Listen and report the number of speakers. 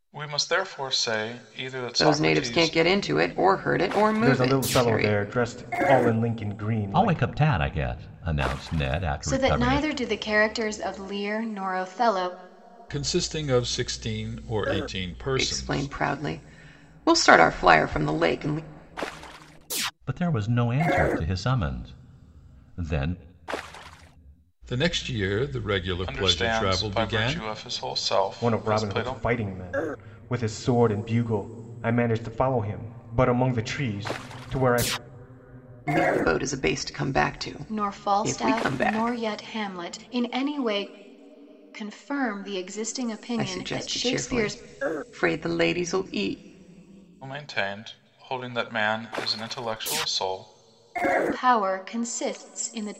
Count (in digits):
6